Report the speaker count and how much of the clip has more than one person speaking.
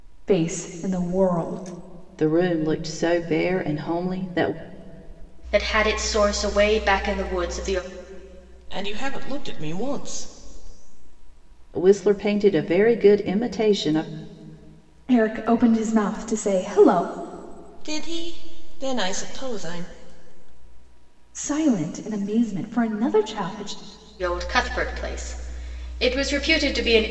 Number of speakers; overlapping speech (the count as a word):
four, no overlap